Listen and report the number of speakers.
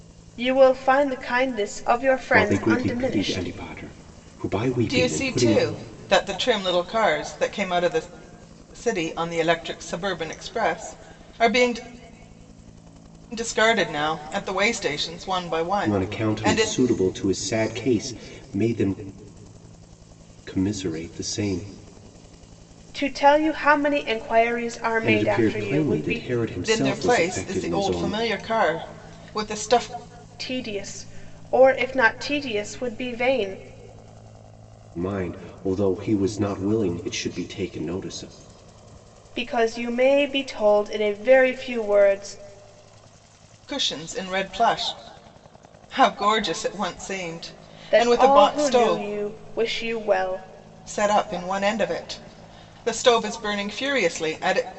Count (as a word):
three